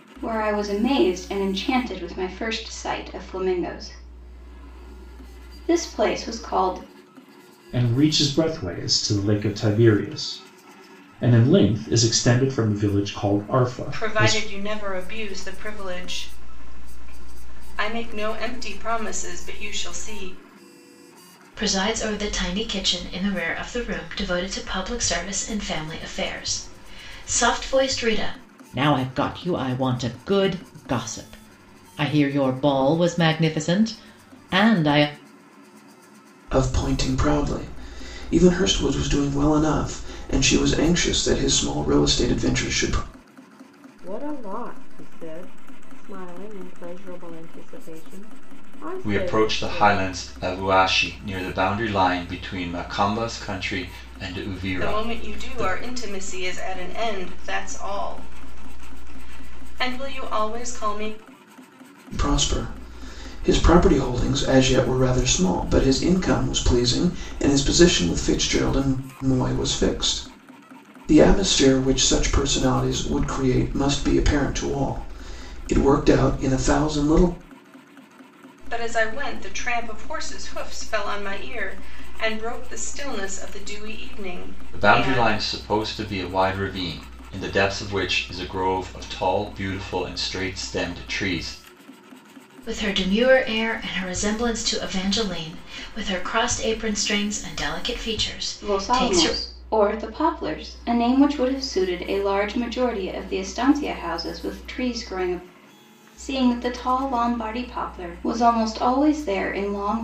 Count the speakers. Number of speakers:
eight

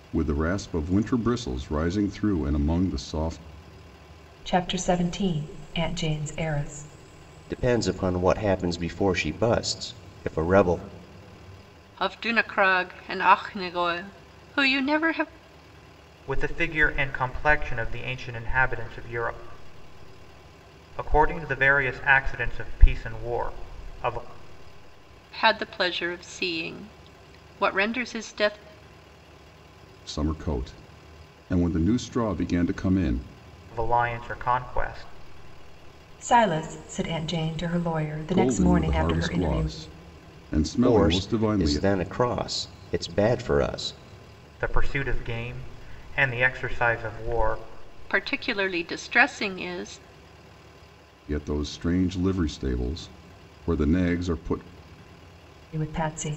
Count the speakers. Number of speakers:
five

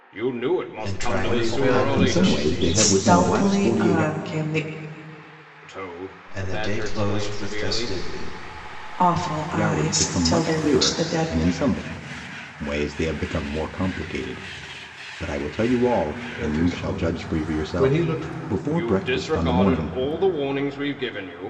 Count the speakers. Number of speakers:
five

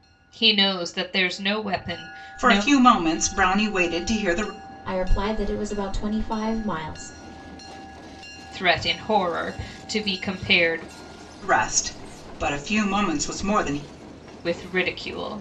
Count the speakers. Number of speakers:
three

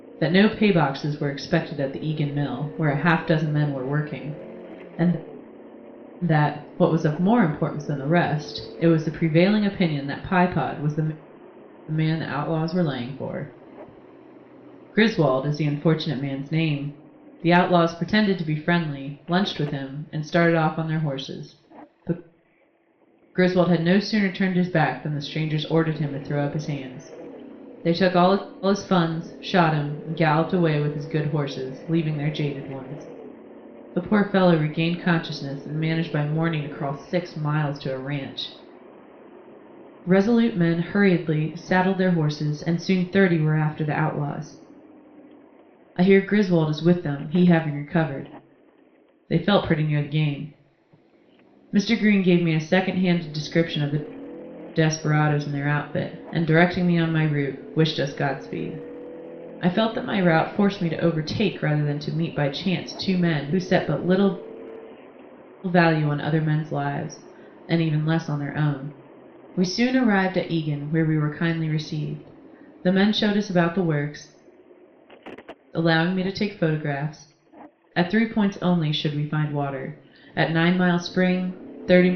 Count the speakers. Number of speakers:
one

